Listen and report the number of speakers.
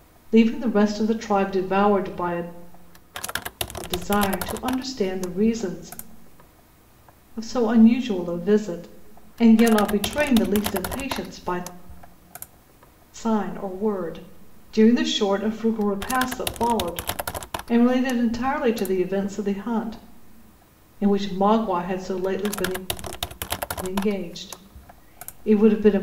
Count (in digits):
1